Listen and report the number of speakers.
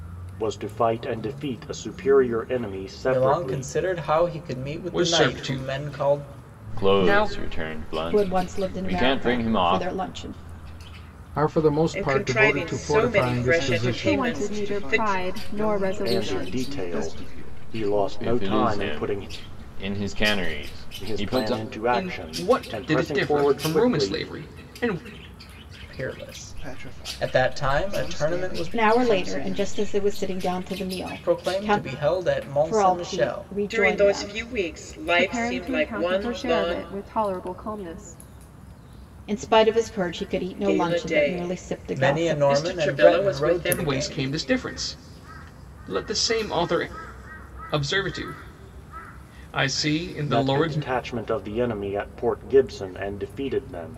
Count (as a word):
nine